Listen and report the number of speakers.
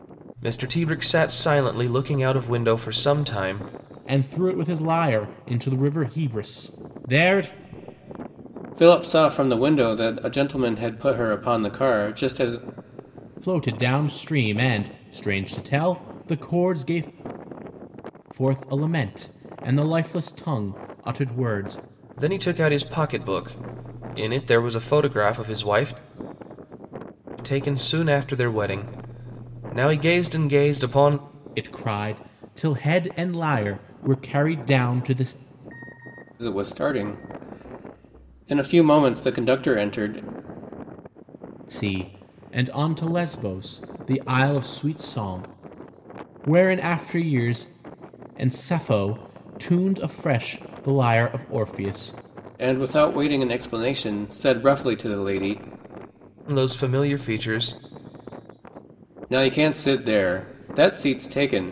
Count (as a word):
three